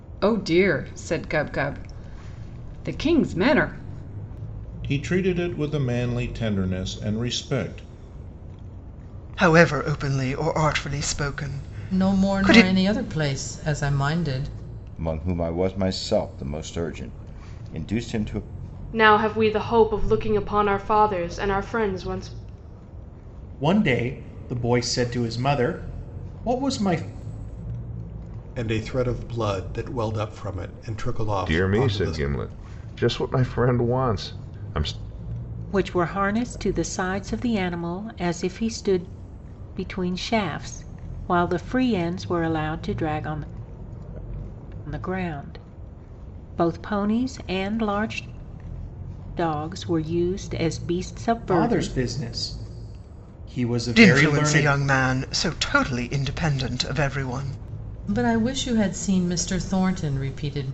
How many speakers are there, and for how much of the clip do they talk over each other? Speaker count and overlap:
10, about 5%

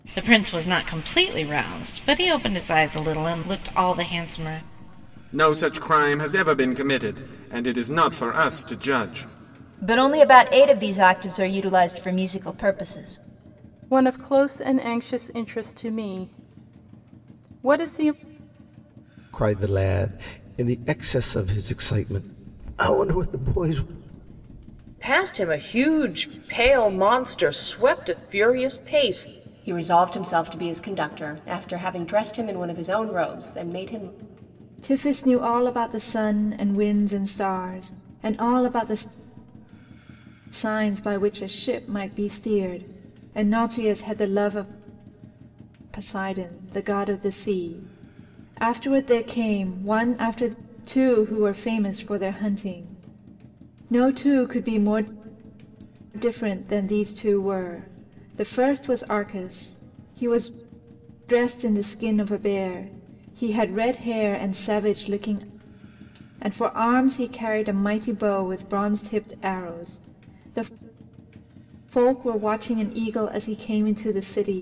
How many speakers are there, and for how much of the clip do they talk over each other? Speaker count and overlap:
8, no overlap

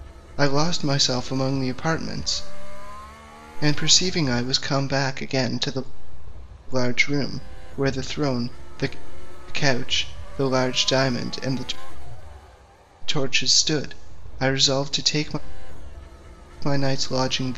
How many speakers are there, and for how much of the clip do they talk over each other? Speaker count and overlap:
1, no overlap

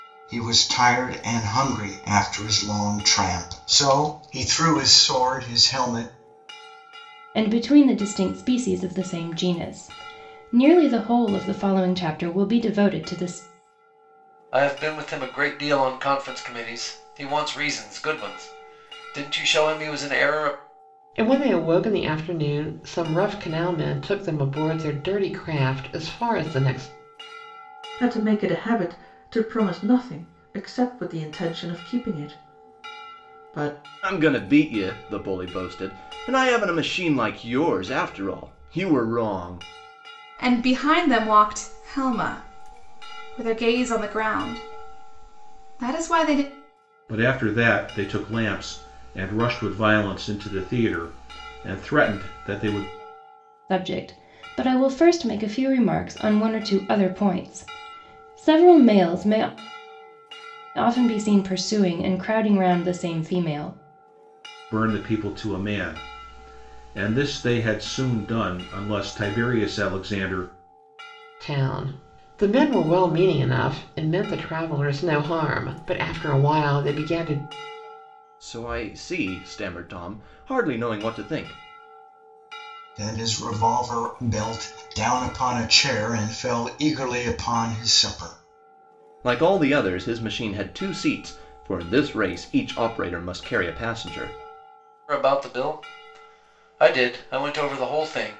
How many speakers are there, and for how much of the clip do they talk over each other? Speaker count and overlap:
8, no overlap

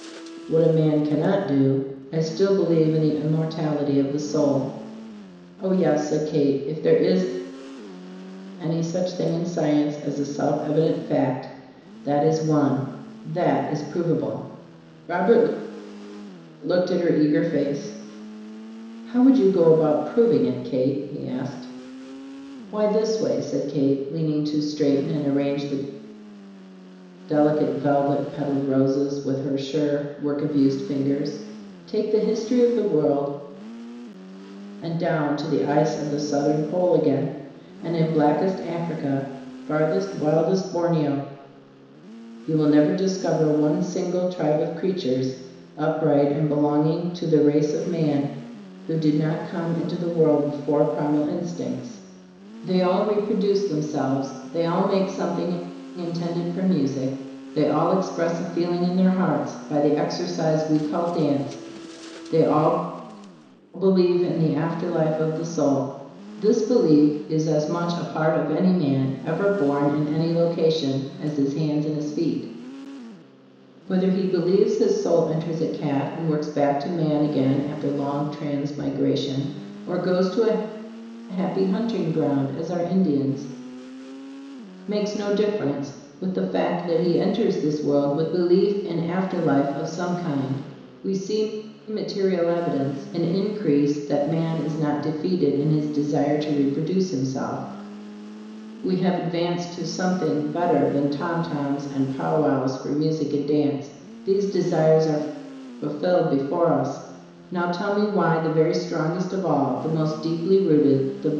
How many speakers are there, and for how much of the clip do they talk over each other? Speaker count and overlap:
1, no overlap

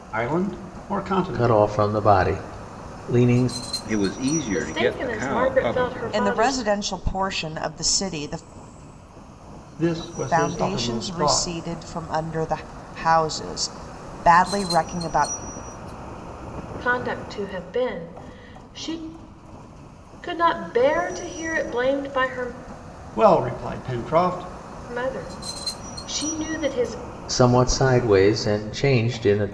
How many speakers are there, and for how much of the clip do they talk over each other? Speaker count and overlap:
5, about 13%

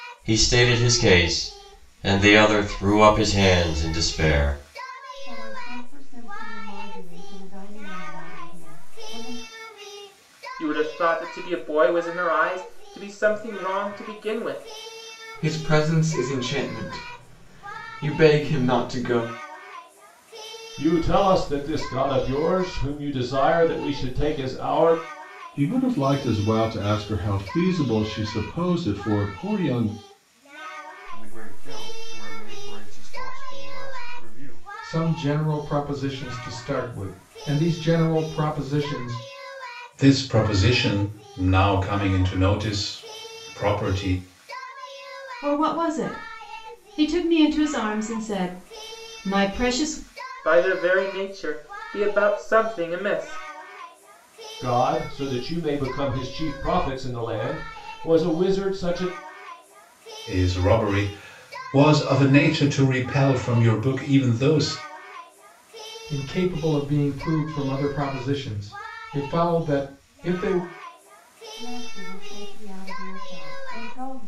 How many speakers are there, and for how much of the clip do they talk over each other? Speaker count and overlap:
10, no overlap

